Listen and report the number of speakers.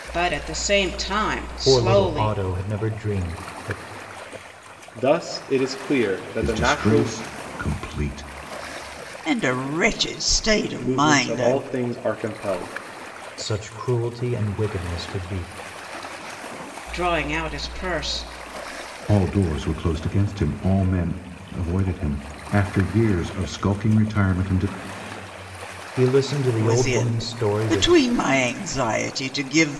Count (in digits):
5